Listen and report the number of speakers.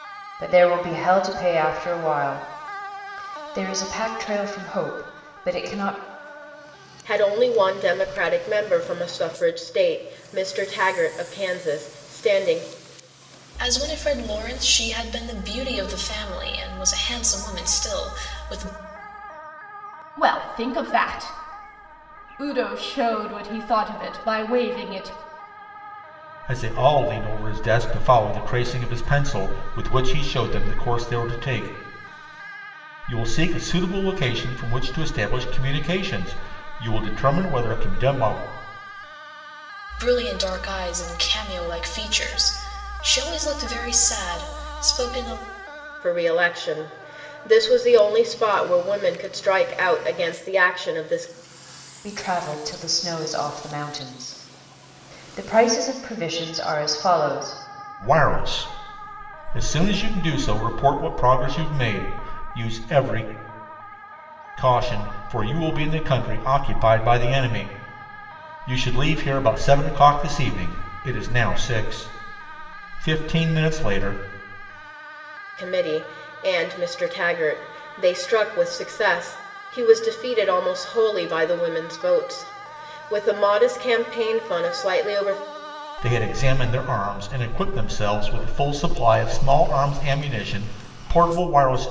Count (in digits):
5